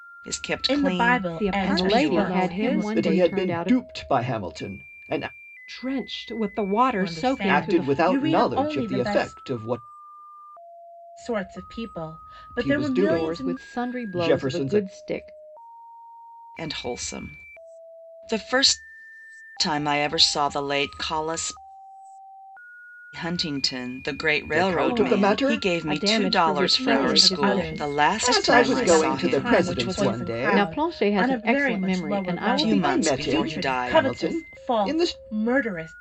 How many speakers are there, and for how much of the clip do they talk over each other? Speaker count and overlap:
five, about 51%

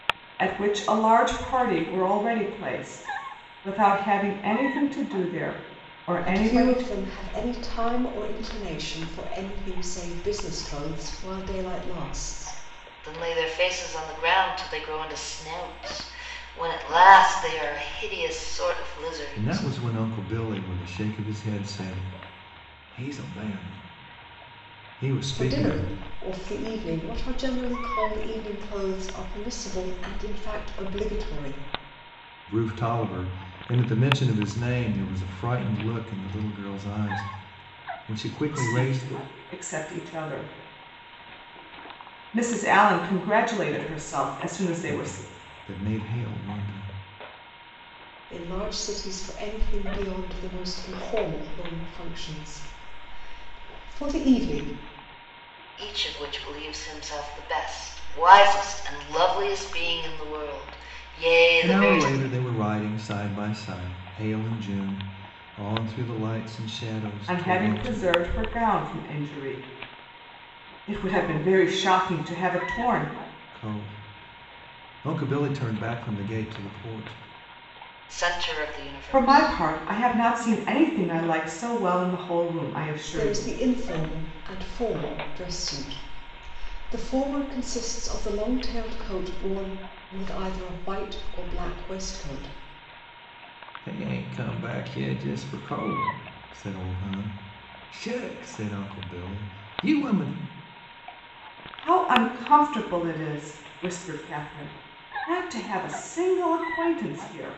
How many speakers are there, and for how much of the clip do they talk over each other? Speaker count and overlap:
four, about 5%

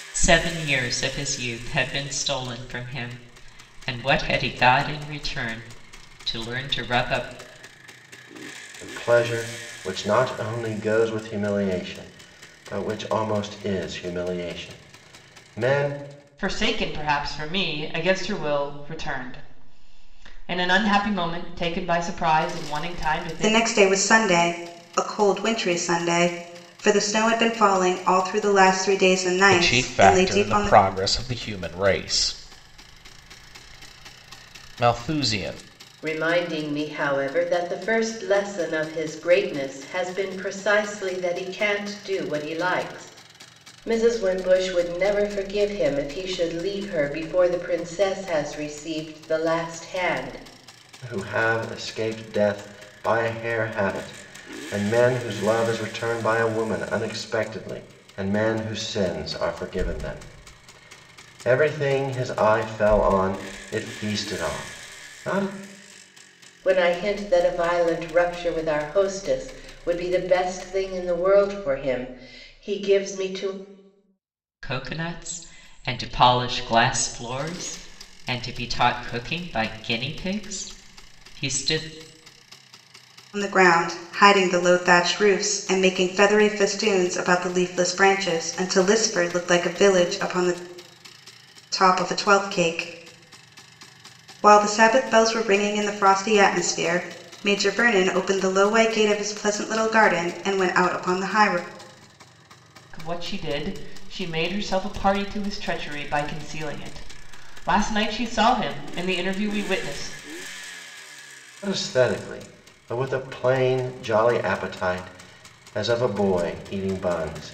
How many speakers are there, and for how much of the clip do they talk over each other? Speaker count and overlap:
six, about 1%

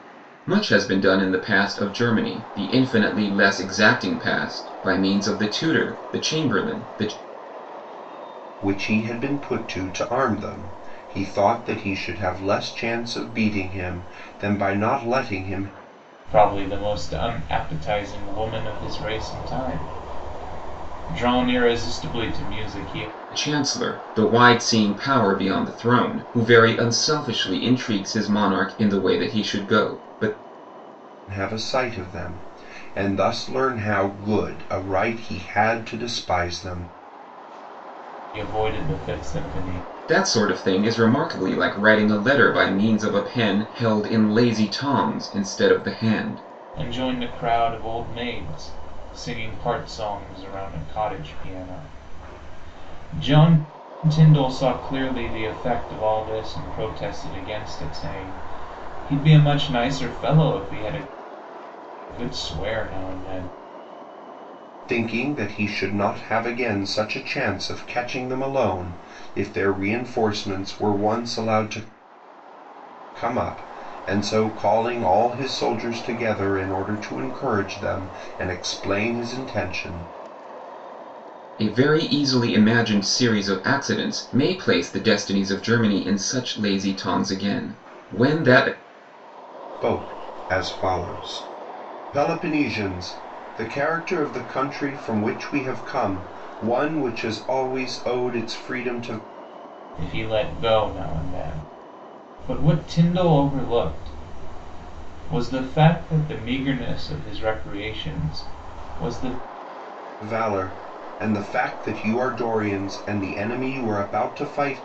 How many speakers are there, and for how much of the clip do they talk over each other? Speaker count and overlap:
three, no overlap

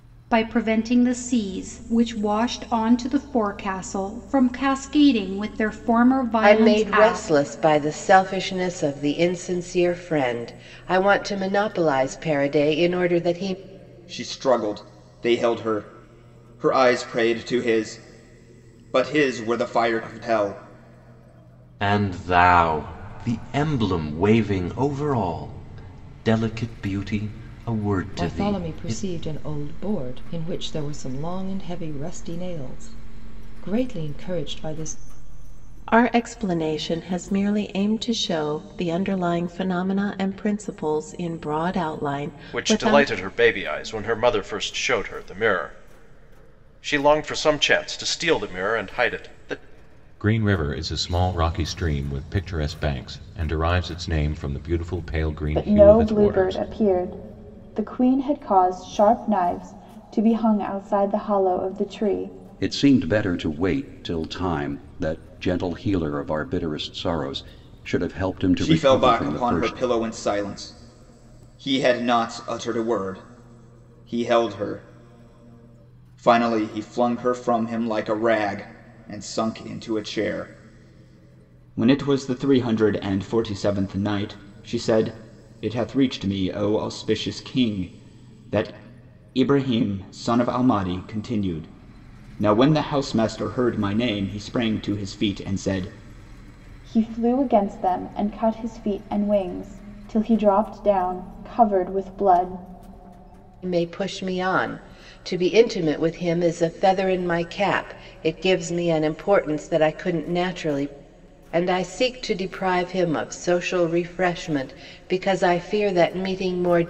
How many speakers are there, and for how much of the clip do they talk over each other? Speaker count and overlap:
ten, about 4%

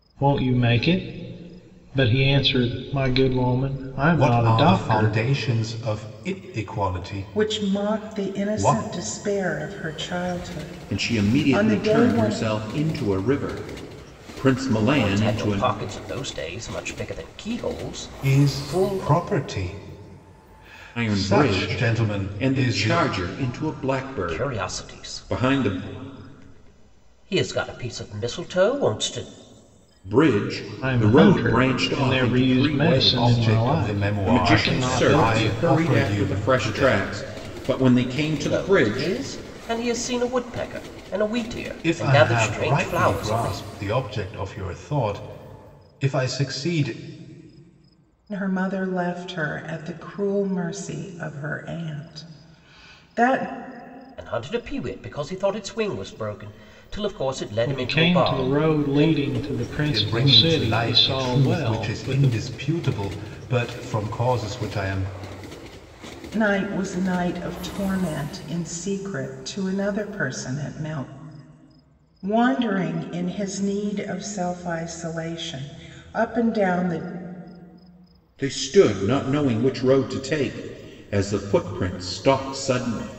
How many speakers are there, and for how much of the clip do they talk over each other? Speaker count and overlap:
five, about 28%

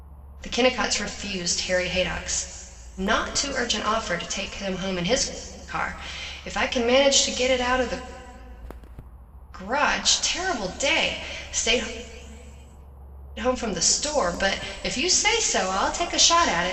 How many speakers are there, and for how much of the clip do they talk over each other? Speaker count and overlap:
one, no overlap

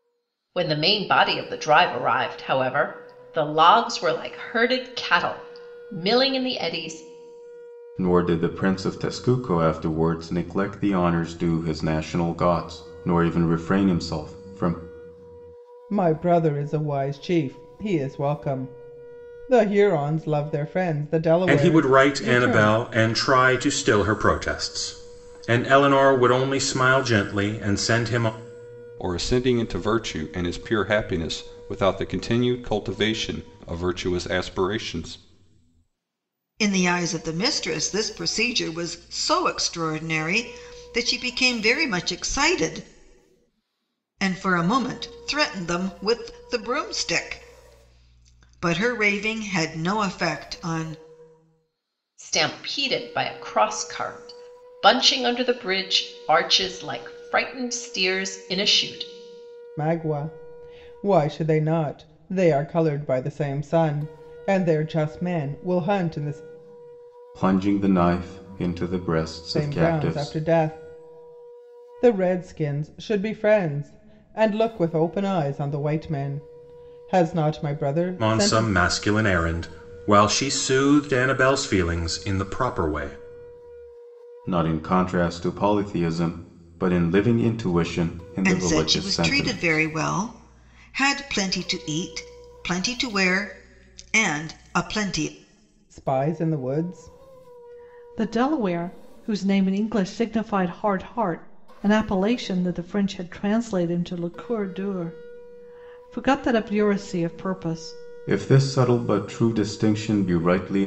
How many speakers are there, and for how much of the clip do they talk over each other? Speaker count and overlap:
six, about 4%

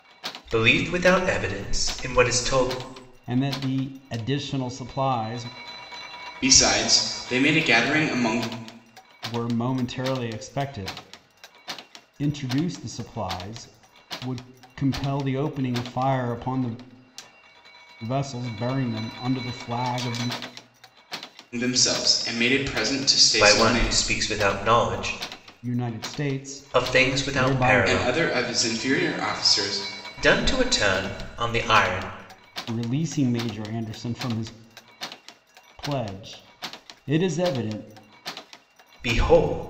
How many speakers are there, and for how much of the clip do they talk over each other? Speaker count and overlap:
three, about 5%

